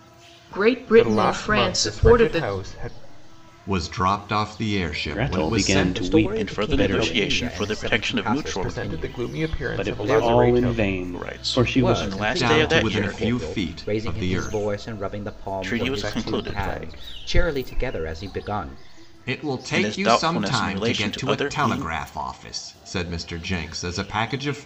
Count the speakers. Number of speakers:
6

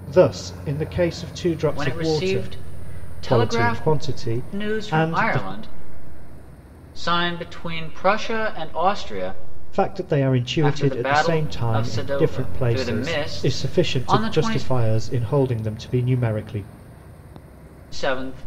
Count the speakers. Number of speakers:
2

